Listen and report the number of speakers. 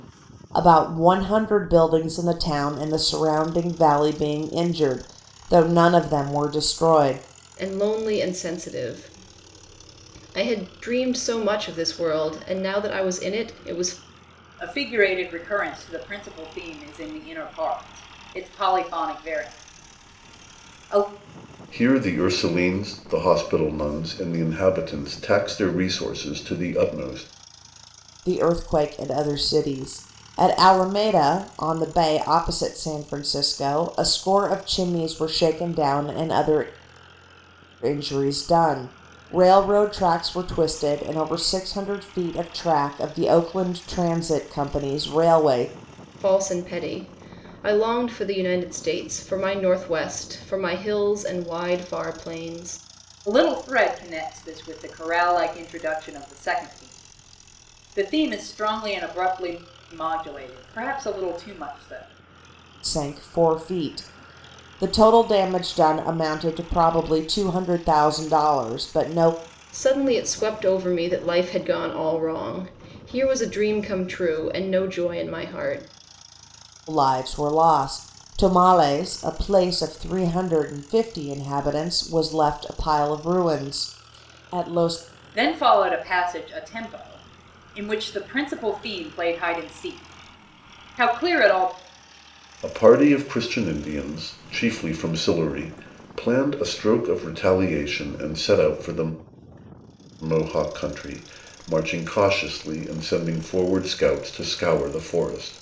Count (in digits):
4